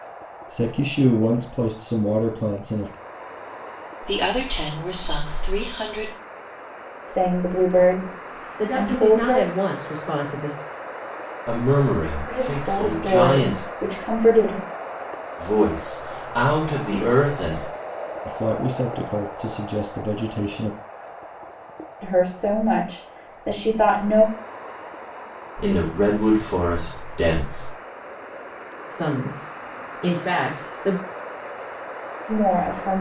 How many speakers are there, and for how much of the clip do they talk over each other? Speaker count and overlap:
5, about 7%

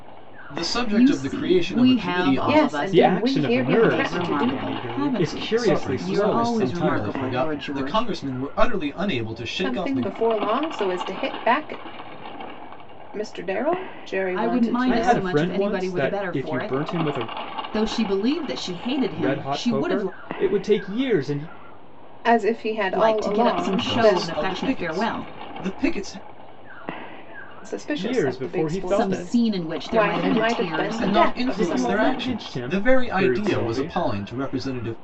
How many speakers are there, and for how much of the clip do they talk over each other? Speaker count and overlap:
4, about 56%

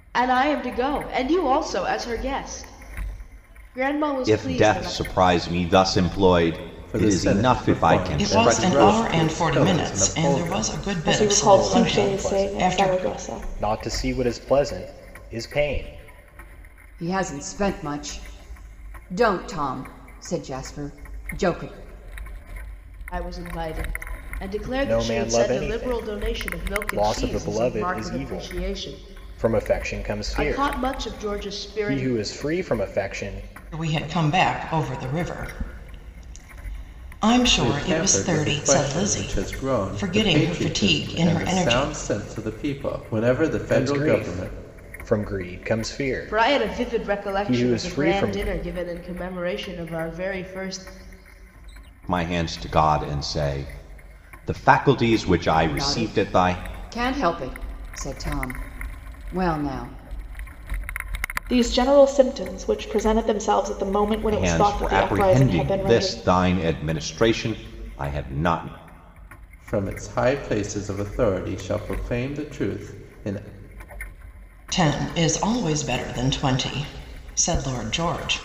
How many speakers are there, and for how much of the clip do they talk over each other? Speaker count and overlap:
7, about 31%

